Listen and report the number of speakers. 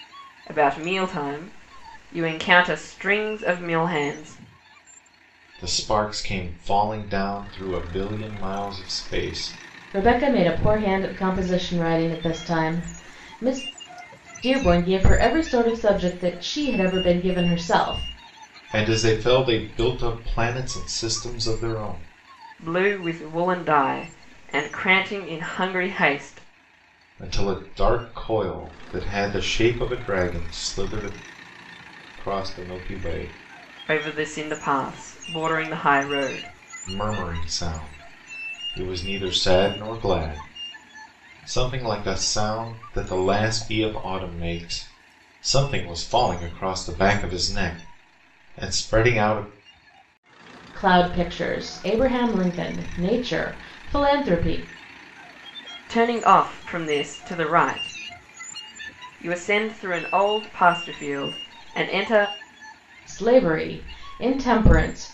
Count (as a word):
three